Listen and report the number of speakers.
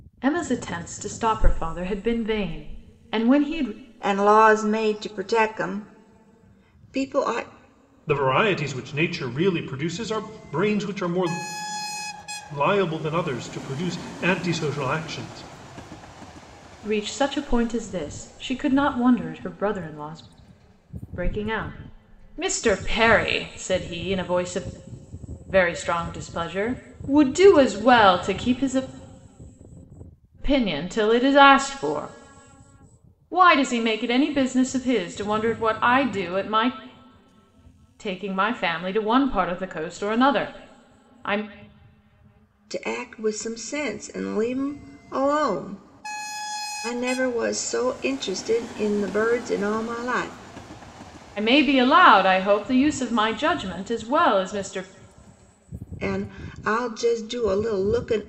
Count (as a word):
three